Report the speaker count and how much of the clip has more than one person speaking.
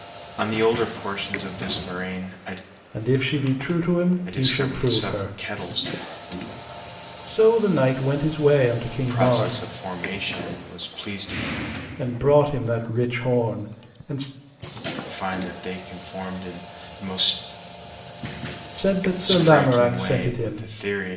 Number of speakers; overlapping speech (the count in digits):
2, about 15%